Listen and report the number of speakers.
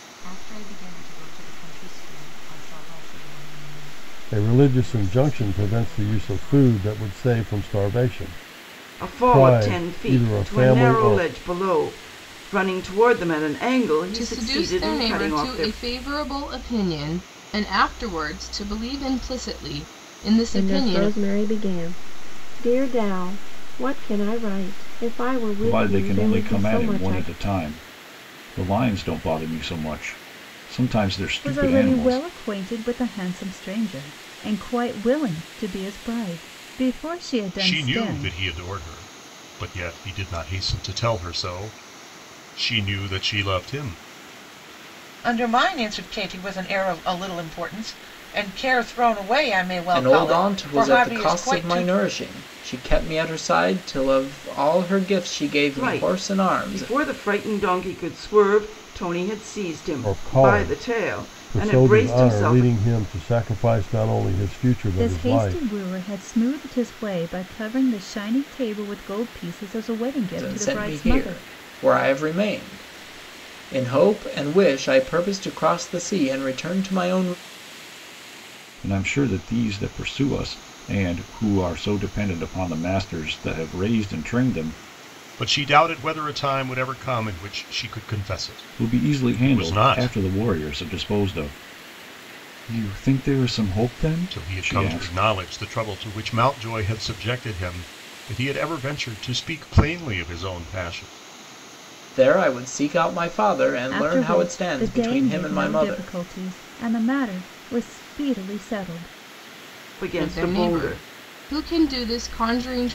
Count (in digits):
10